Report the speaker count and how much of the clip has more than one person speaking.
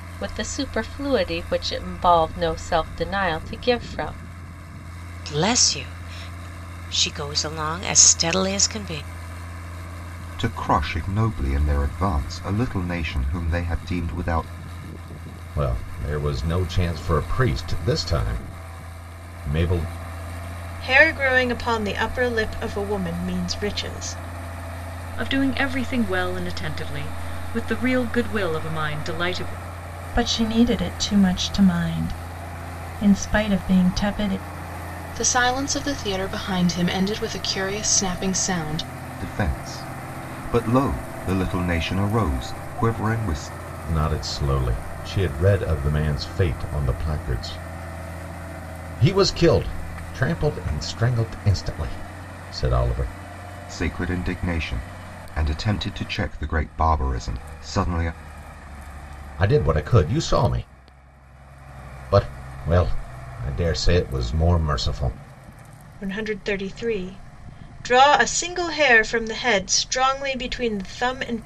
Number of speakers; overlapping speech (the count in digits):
8, no overlap